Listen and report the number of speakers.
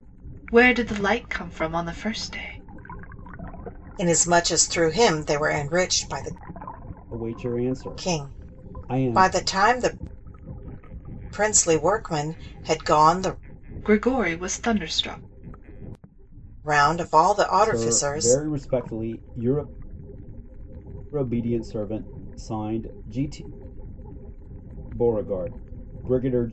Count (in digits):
3